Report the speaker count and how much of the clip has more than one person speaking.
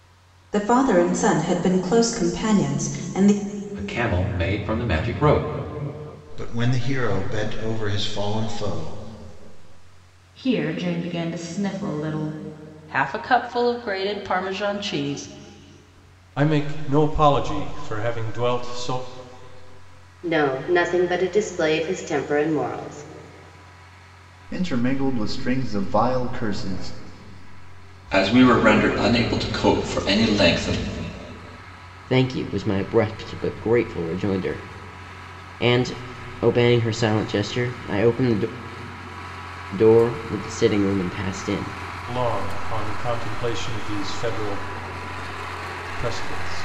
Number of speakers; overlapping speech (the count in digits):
10, no overlap